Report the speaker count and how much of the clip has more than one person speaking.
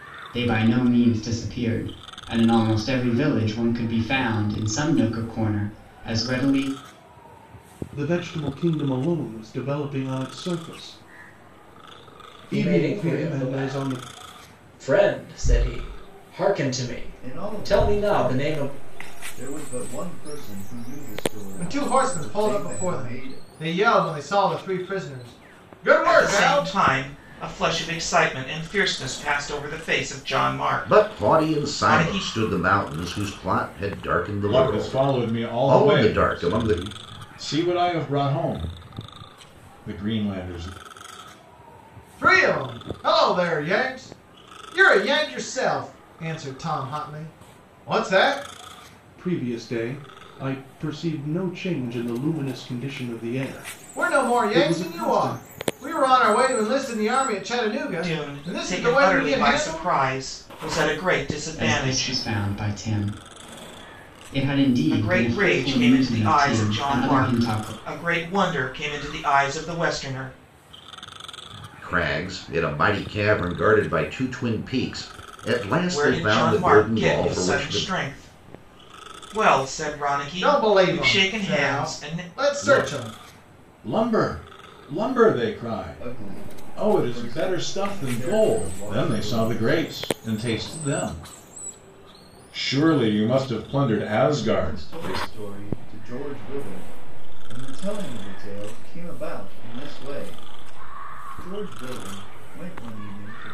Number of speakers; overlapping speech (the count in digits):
8, about 25%